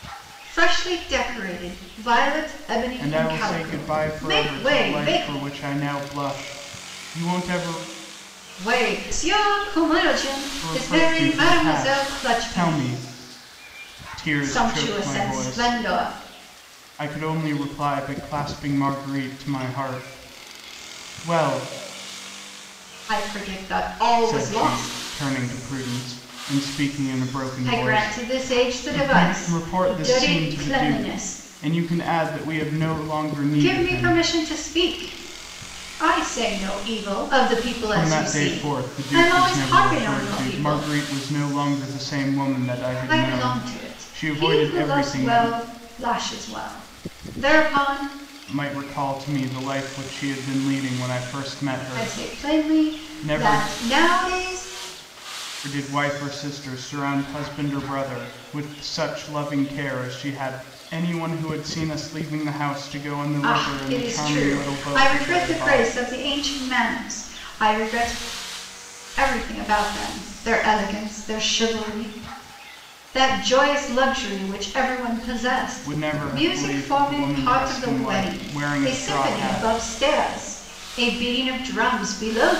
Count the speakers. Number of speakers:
2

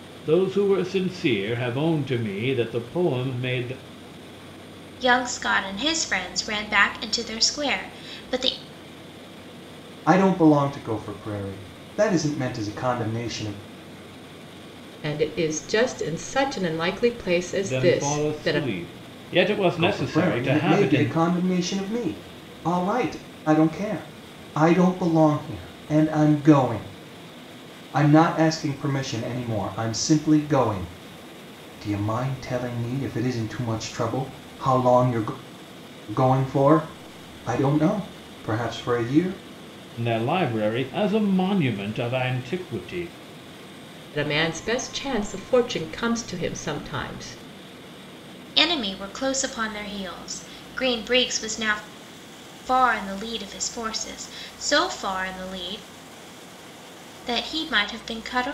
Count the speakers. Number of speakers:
4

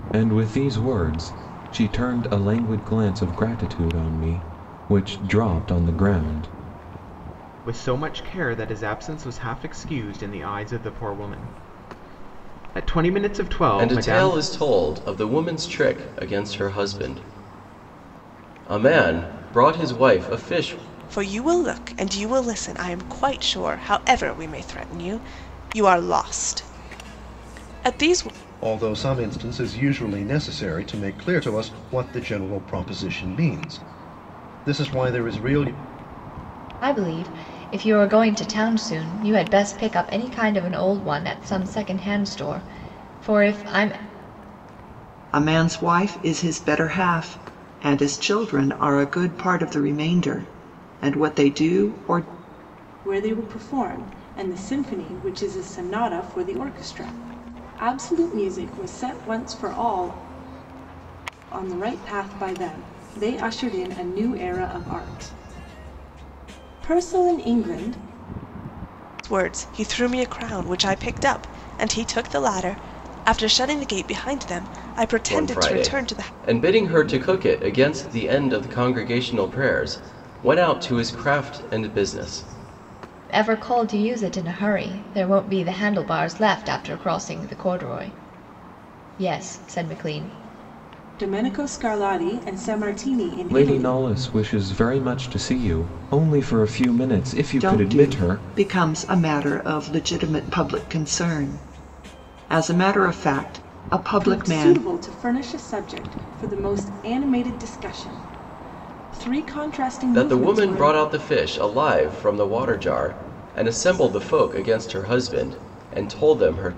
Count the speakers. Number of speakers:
8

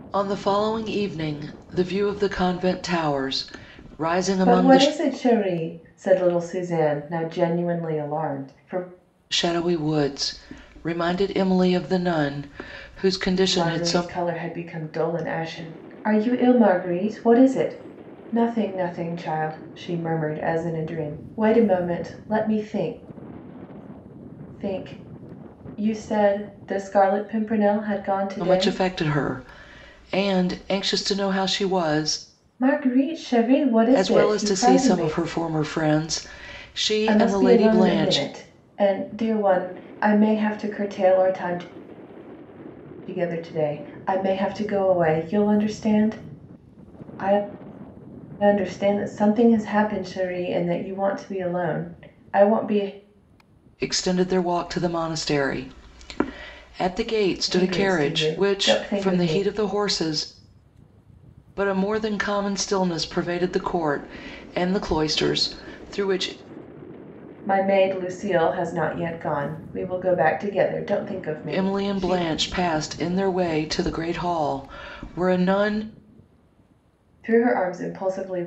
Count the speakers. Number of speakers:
2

